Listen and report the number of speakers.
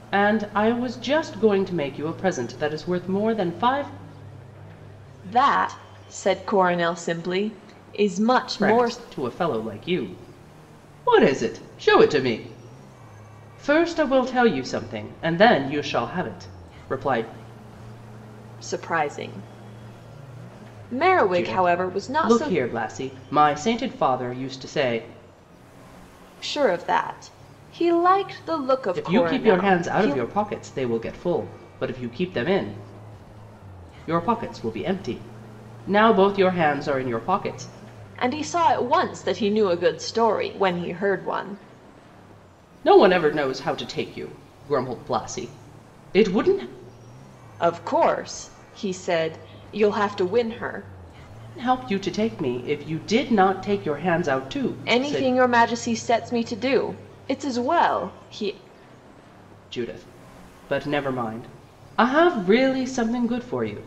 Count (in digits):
2